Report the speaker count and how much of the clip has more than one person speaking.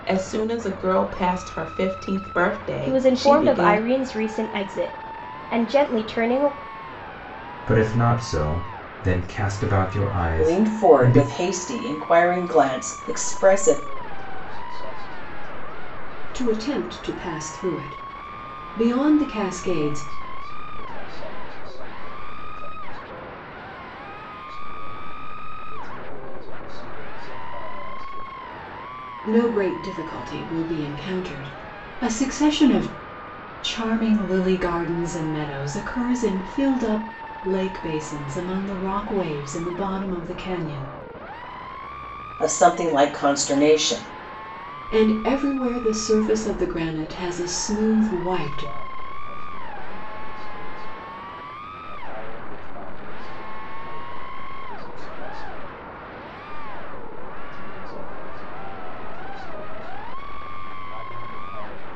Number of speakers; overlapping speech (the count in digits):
6, about 6%